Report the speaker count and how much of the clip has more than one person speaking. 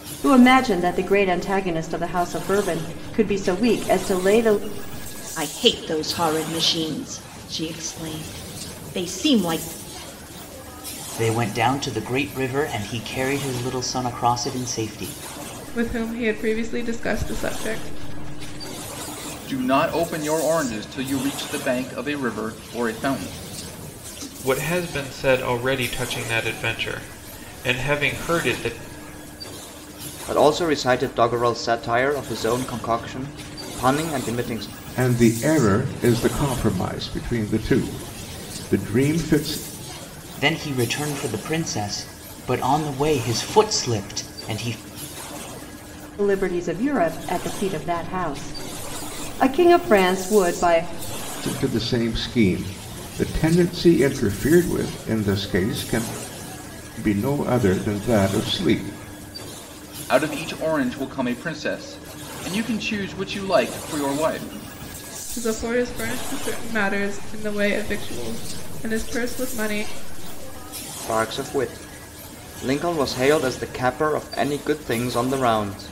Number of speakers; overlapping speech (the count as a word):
eight, no overlap